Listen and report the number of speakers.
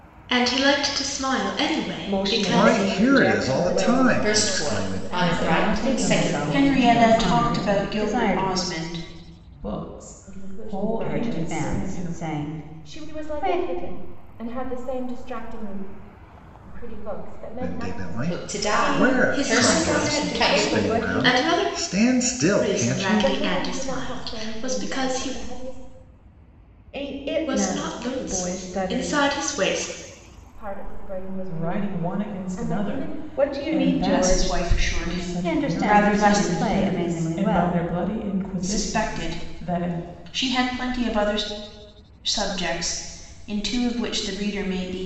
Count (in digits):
8